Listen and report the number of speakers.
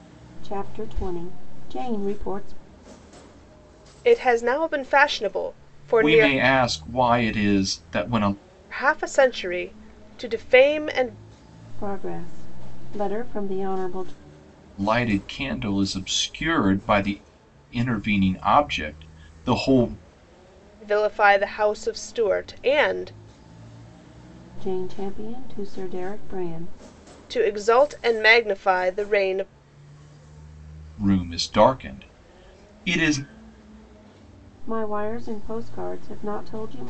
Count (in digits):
3